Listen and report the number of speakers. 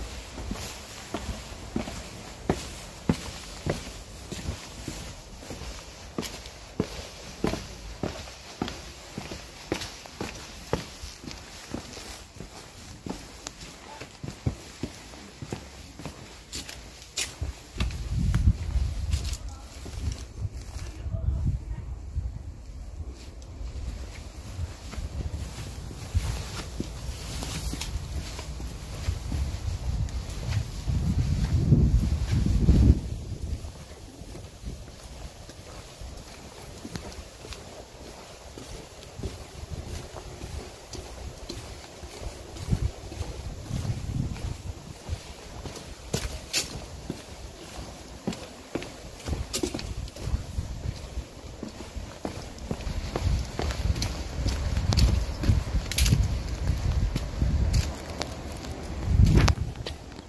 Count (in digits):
0